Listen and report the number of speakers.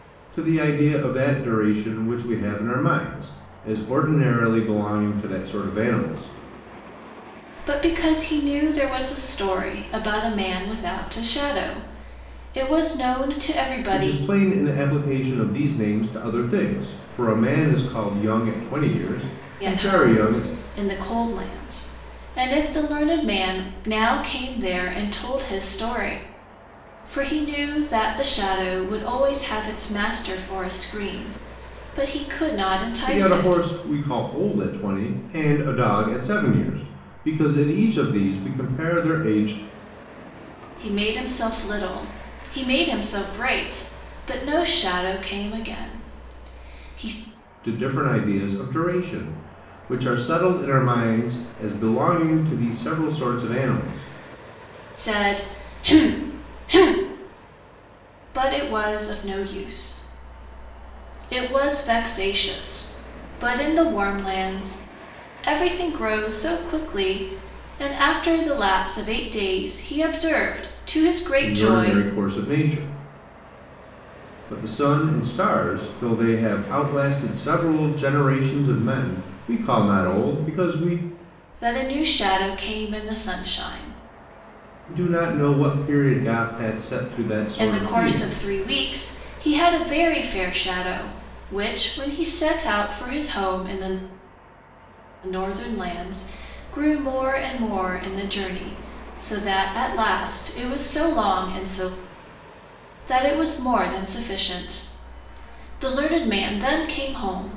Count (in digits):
2